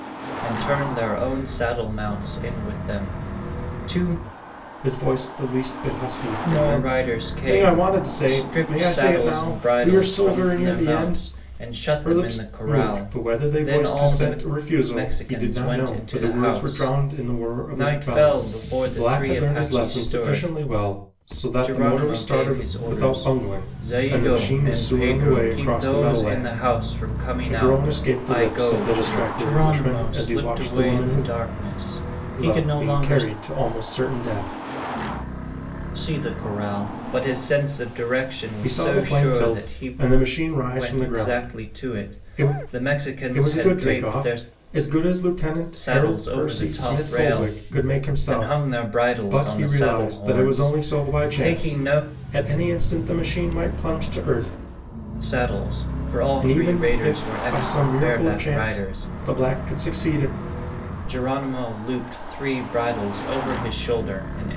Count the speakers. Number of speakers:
two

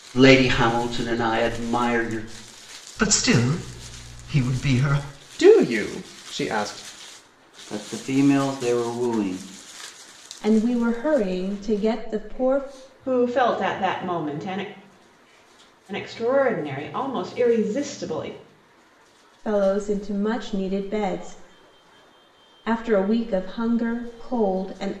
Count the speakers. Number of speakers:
six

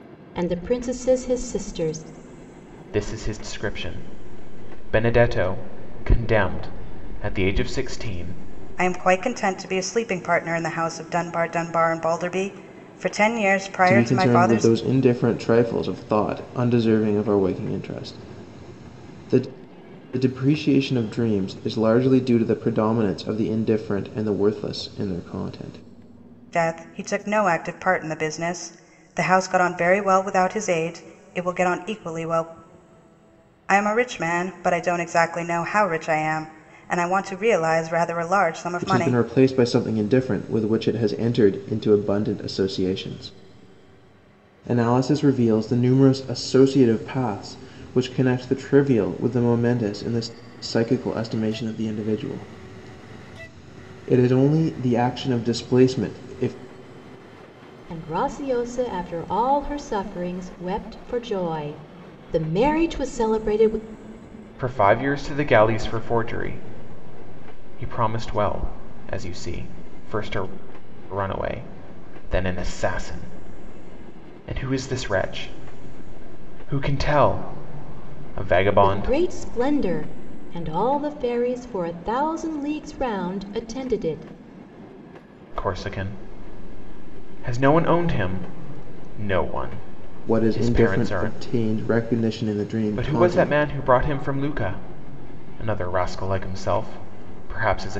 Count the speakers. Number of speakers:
four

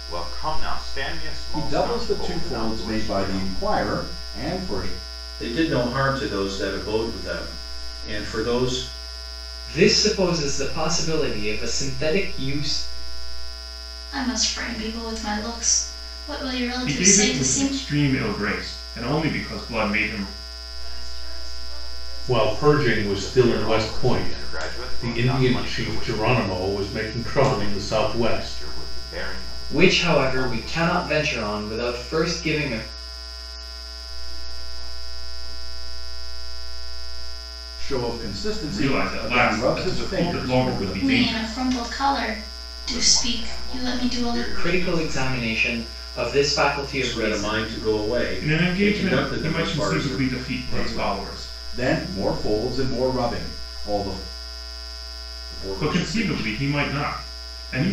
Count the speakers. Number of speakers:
nine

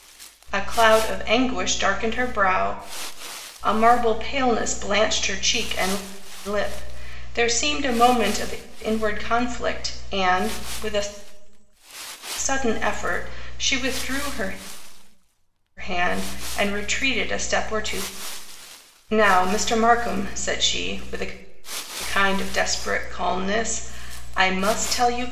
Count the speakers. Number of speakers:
one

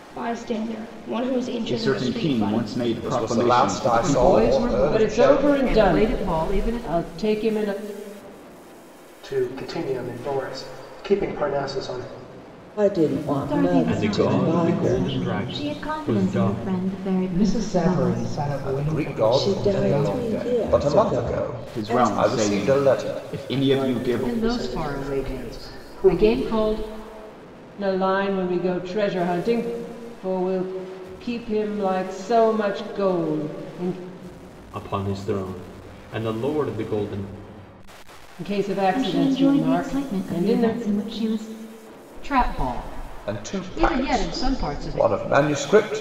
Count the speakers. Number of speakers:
nine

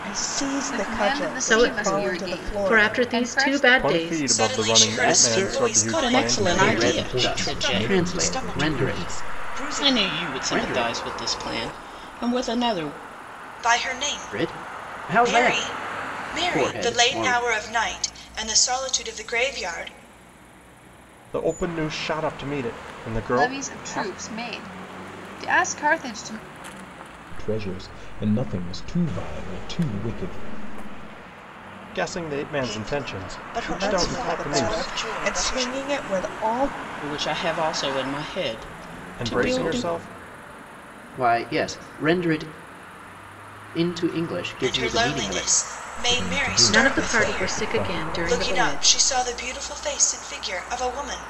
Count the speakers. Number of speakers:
nine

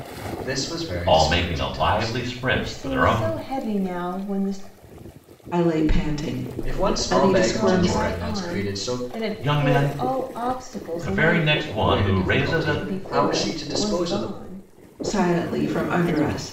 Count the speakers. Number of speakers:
four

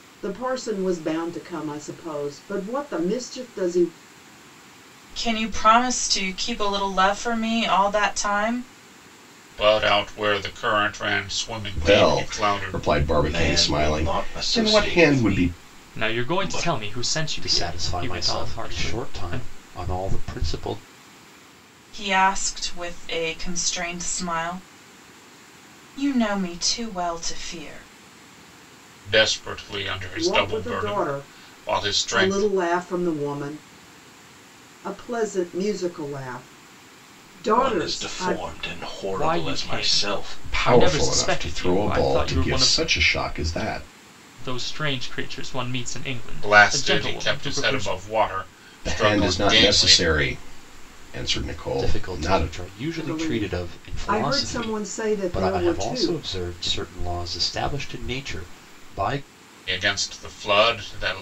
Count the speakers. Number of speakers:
seven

